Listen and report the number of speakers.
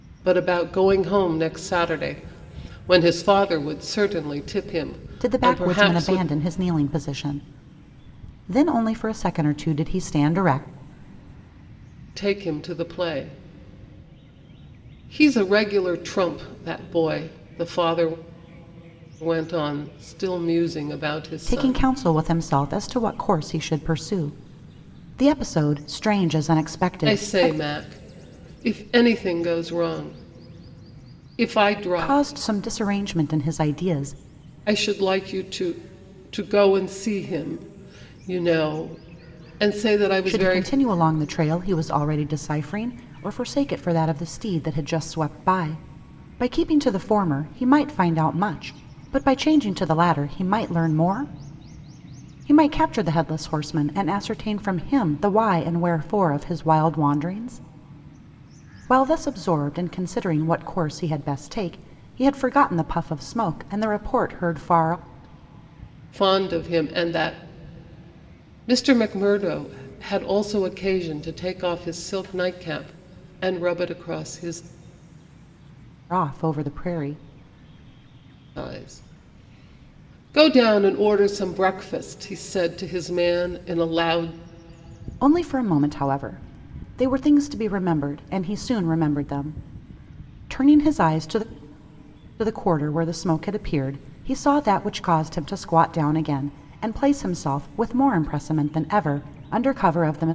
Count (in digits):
2